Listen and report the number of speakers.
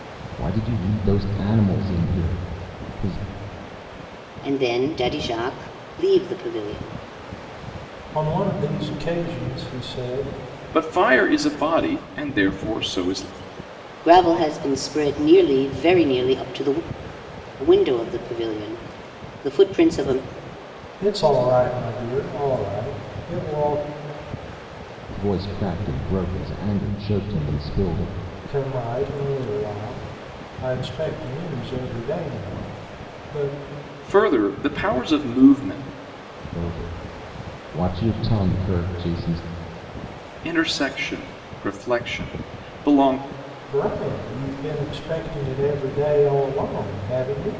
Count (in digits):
4